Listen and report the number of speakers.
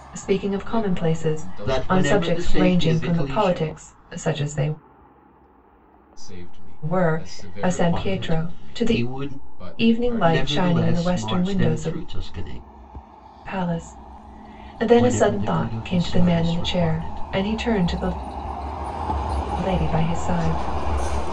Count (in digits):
3